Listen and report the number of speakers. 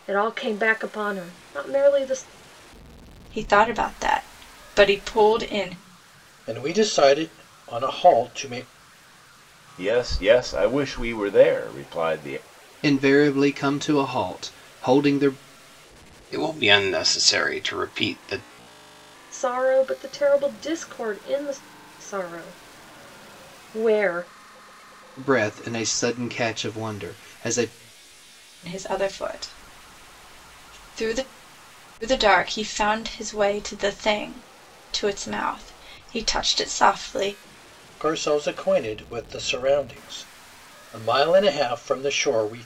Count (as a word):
six